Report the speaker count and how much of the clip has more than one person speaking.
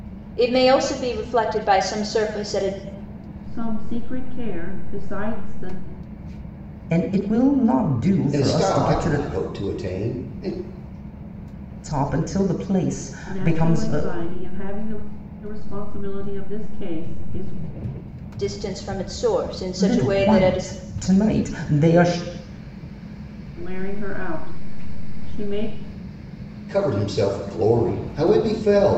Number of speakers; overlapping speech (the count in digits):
4, about 9%